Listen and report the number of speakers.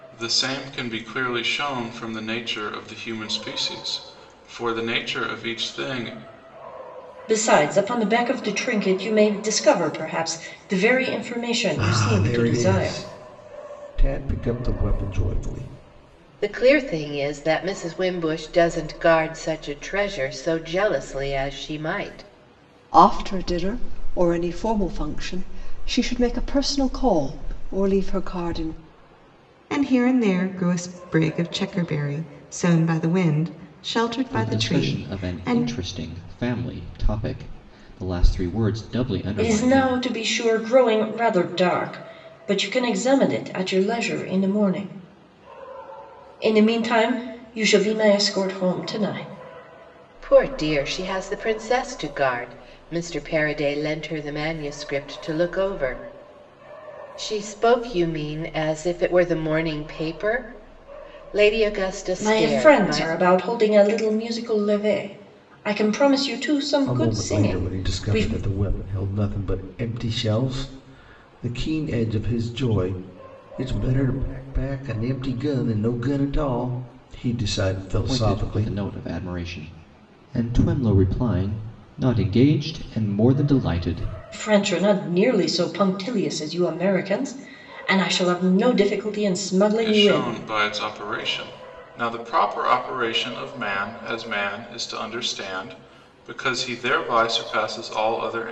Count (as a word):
seven